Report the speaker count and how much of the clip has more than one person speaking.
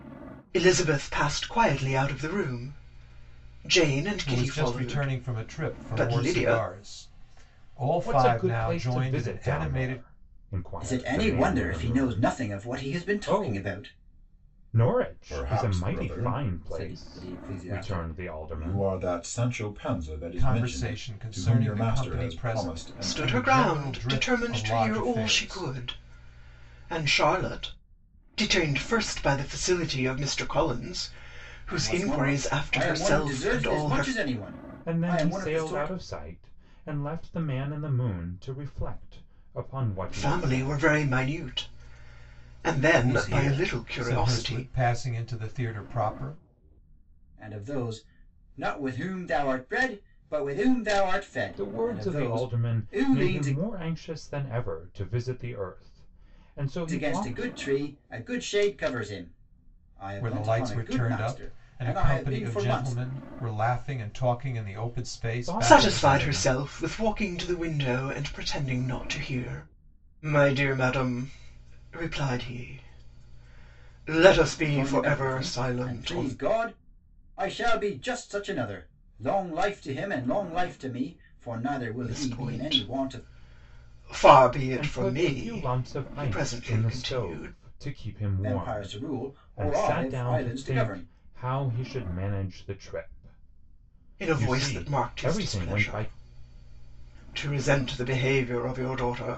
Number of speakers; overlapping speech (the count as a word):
four, about 40%